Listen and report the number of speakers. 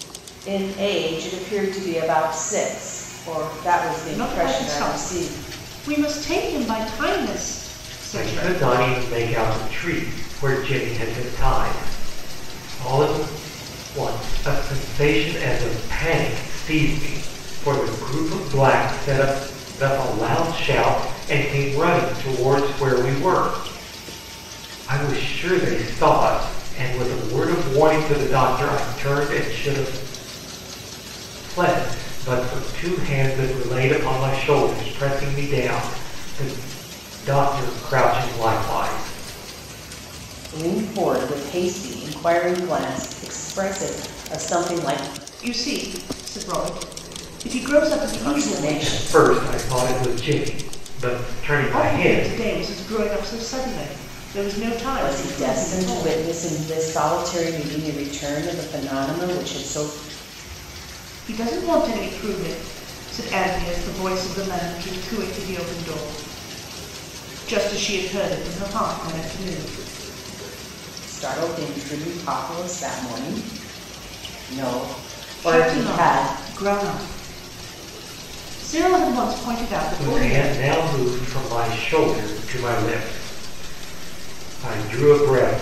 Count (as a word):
three